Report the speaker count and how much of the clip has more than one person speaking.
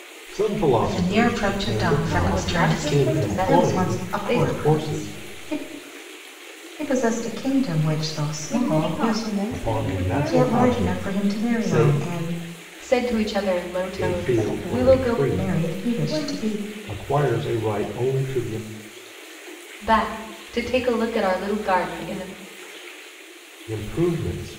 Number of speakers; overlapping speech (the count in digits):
4, about 41%